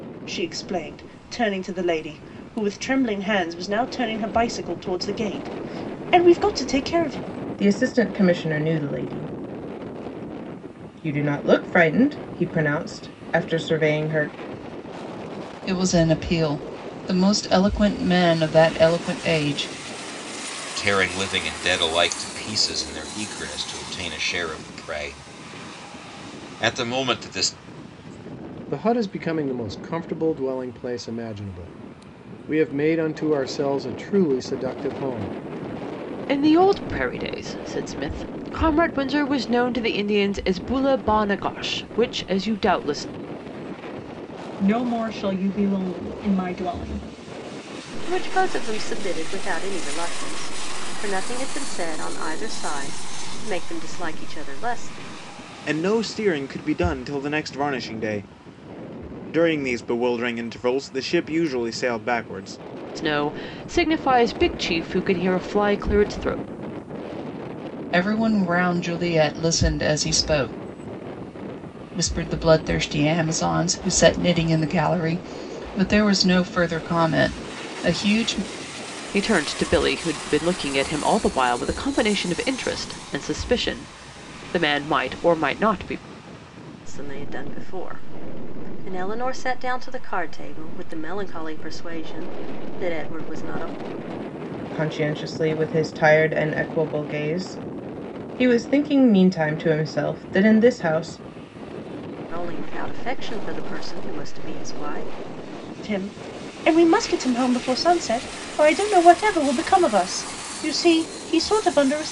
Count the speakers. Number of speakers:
9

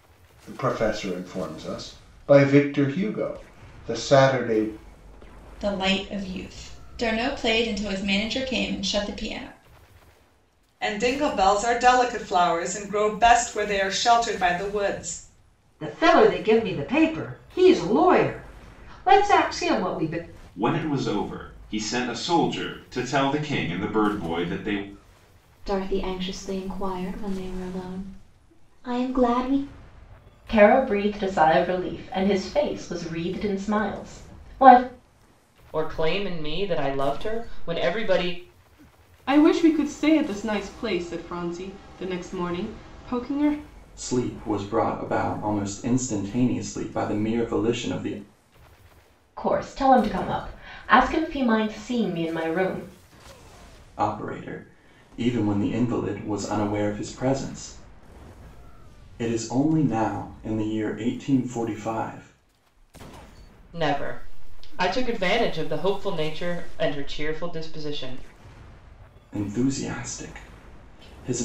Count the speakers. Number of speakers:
10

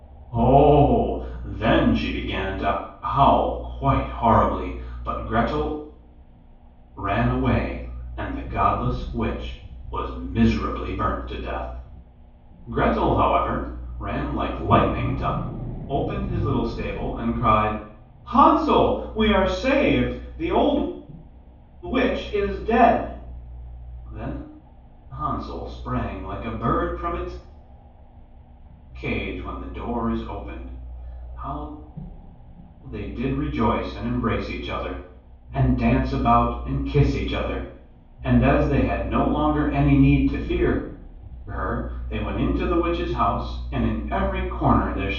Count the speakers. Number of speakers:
1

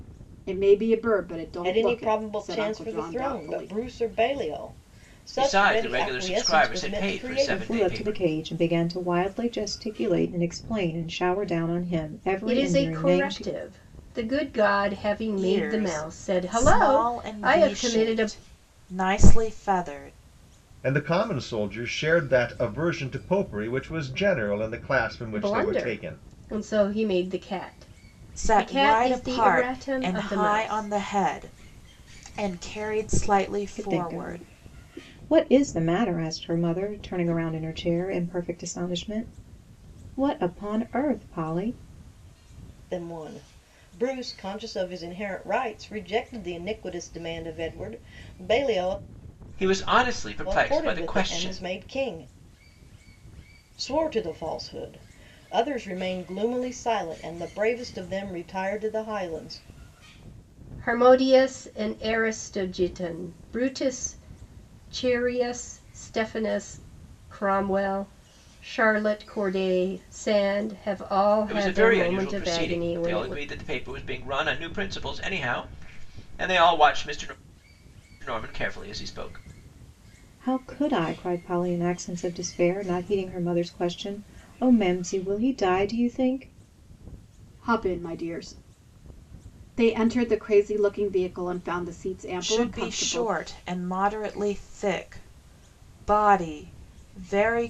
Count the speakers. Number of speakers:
7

